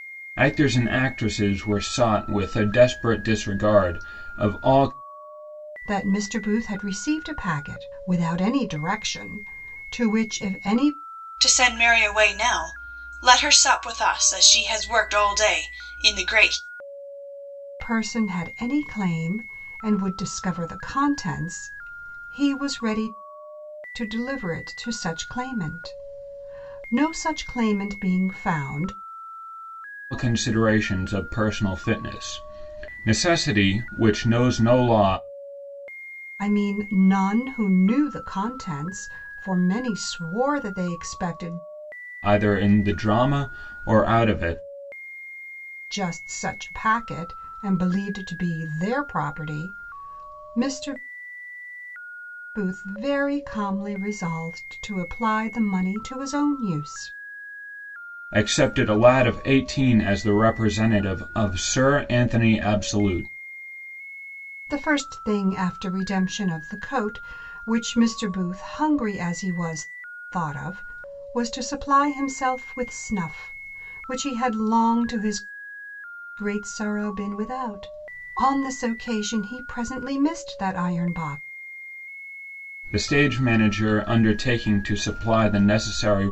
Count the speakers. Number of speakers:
3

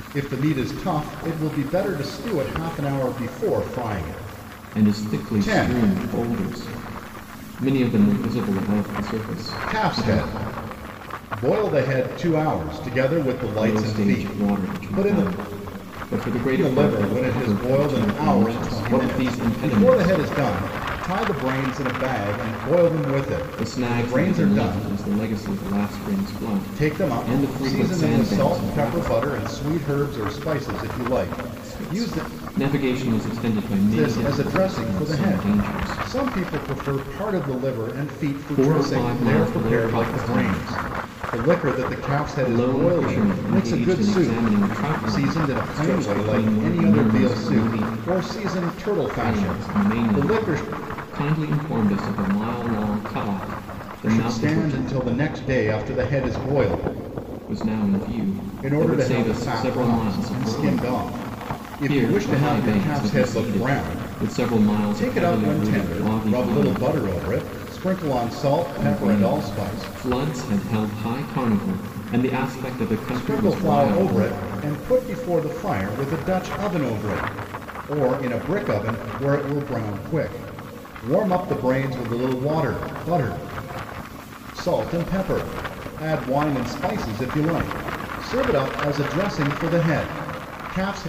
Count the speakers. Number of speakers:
2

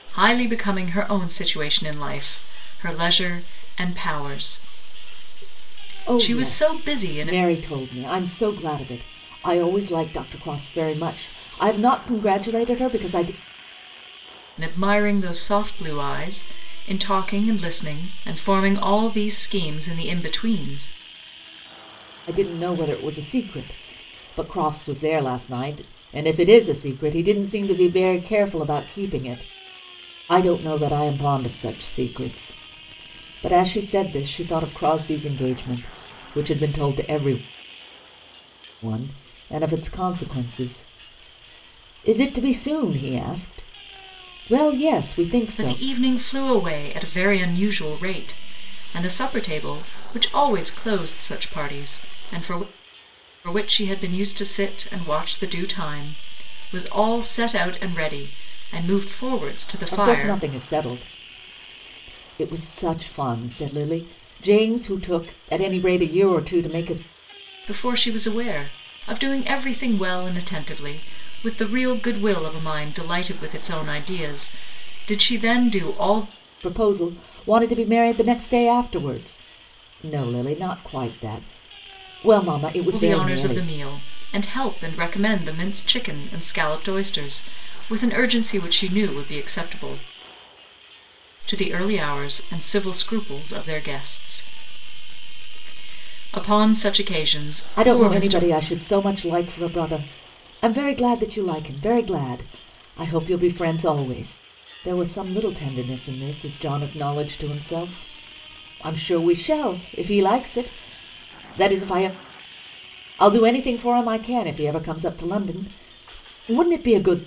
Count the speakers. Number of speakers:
2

